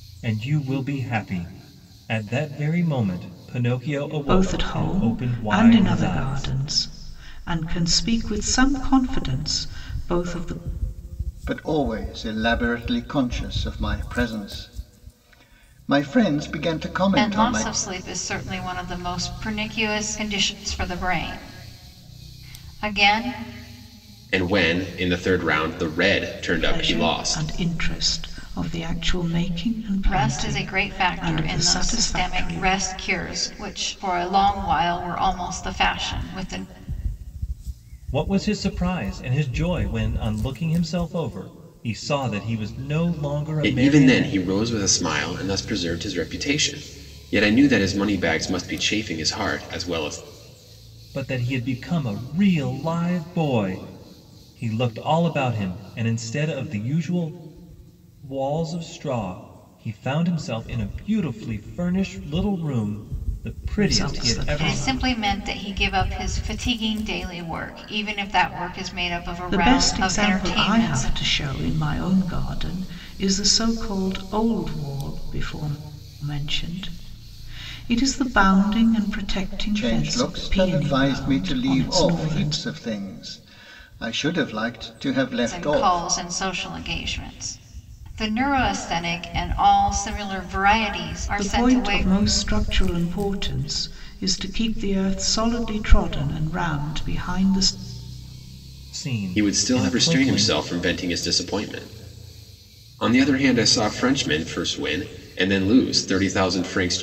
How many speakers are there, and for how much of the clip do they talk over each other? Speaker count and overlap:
5, about 15%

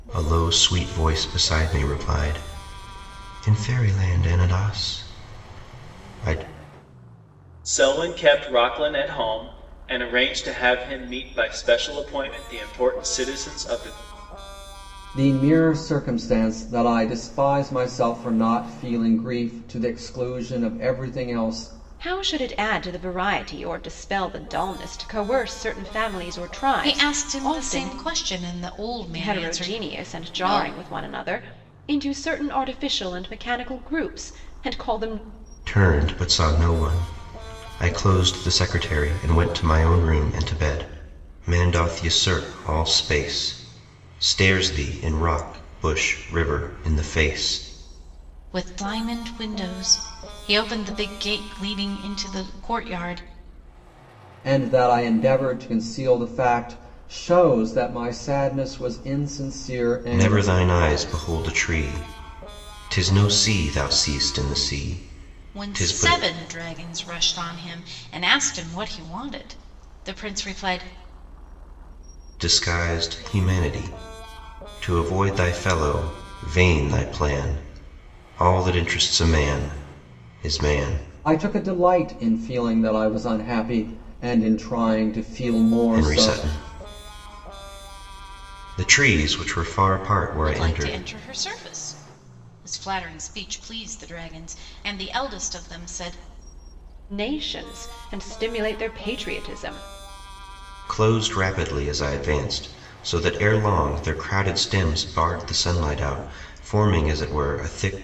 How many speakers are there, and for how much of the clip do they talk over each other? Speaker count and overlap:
5, about 5%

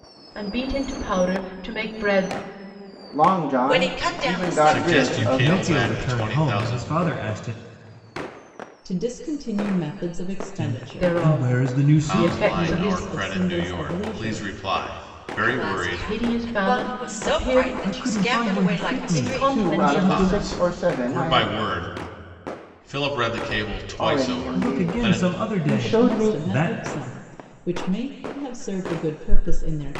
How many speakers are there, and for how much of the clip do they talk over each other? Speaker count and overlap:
6, about 54%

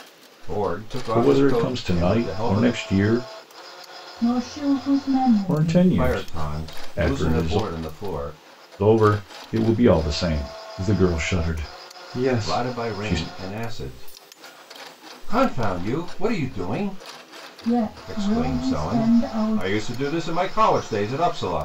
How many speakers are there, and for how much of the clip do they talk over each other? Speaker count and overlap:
3, about 30%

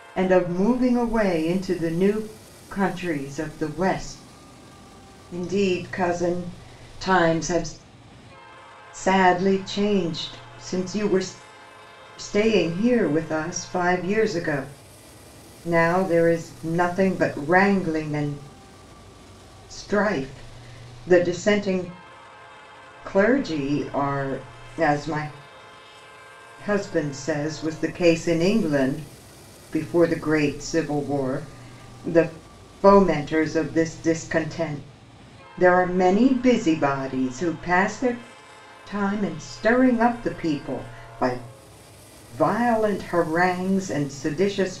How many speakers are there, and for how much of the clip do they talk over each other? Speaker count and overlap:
1, no overlap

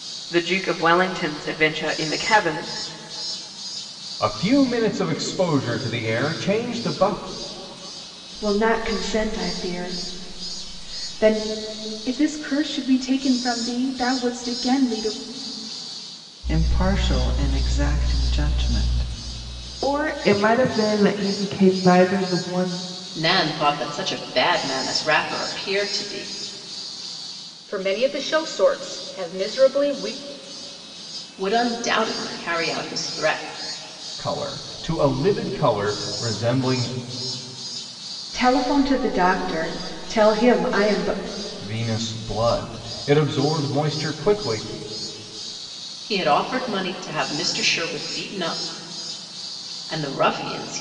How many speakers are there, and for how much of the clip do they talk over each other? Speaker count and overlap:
8, no overlap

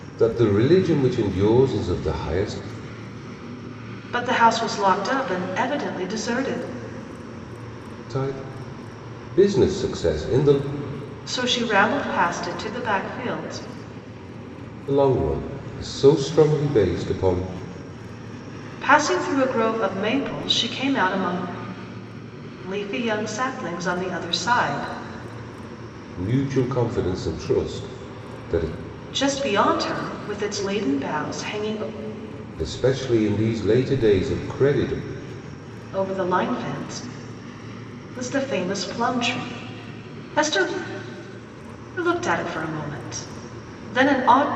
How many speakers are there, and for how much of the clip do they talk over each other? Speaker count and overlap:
2, no overlap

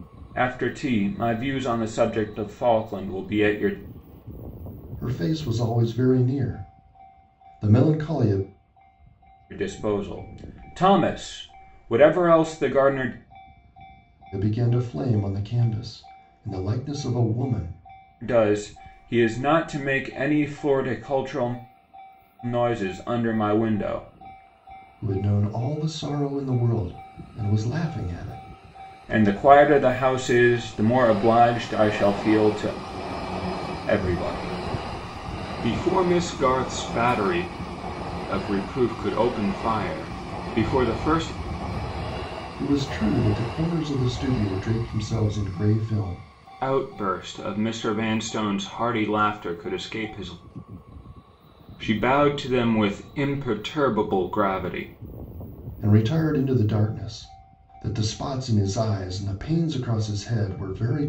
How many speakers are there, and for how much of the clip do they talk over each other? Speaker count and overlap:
2, no overlap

